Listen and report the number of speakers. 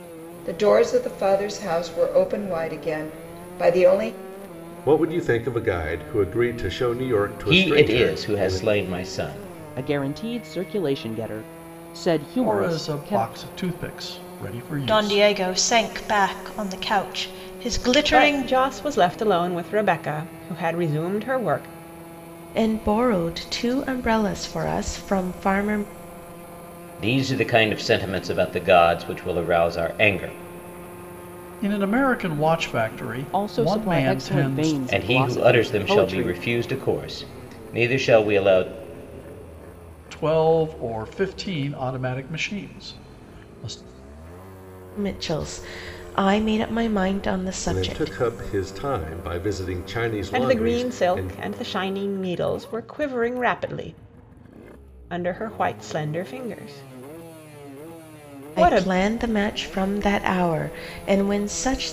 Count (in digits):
8